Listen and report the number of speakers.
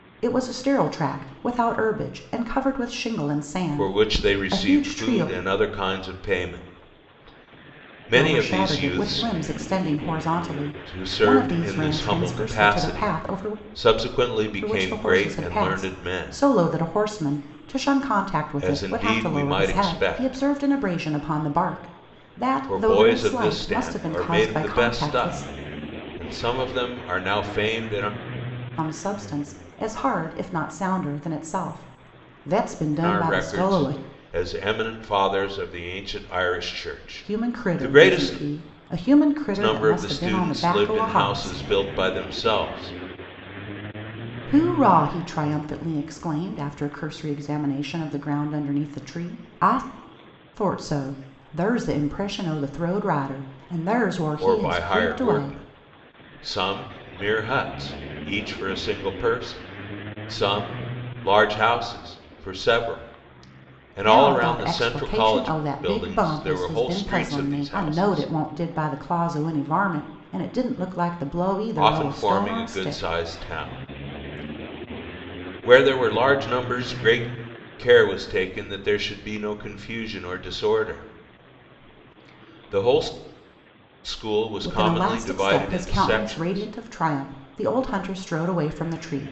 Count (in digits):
2